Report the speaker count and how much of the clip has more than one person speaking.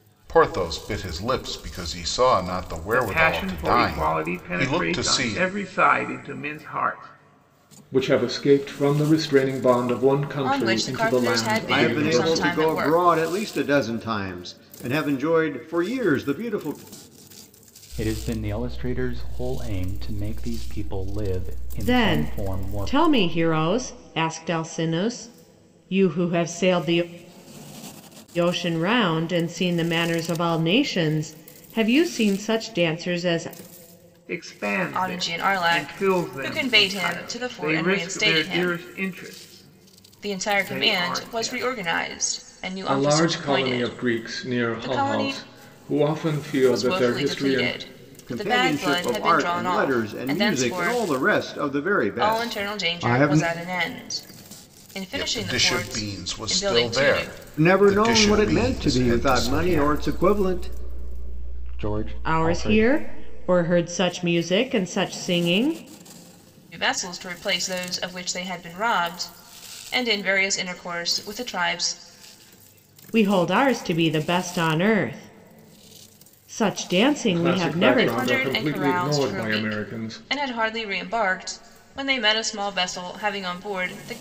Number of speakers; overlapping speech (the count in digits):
7, about 34%